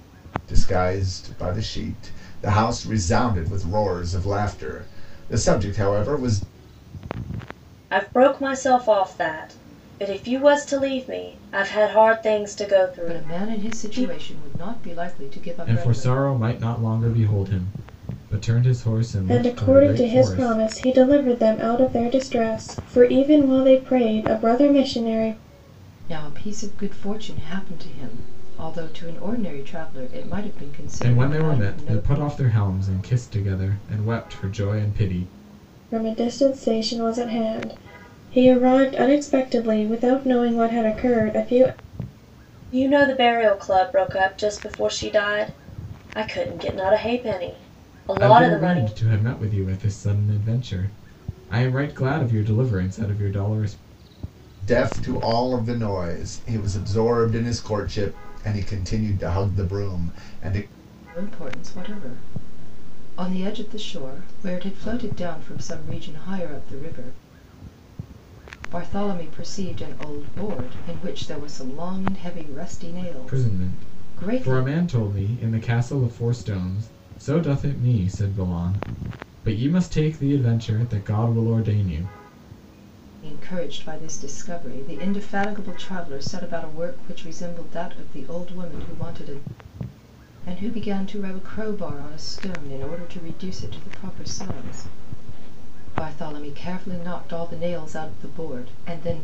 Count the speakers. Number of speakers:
5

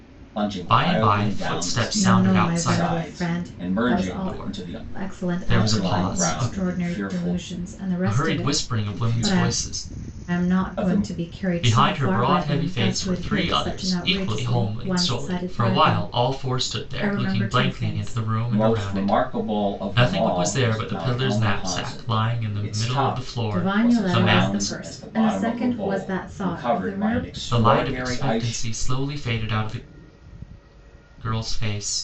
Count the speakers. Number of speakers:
3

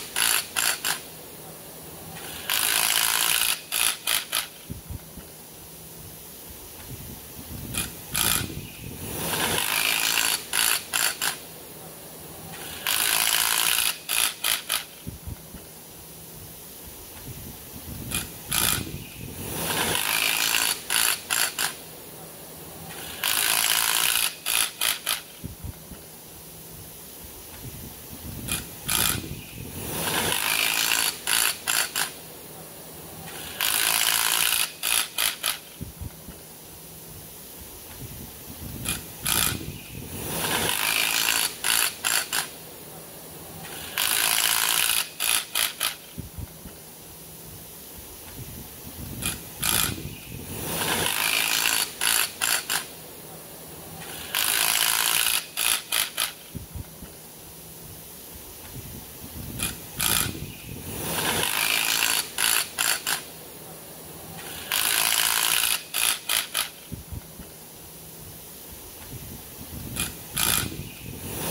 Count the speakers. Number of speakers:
0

